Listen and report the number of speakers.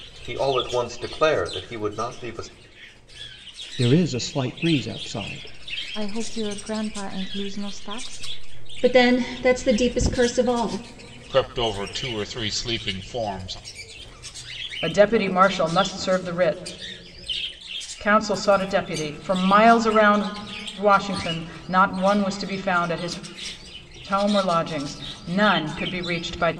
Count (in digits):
6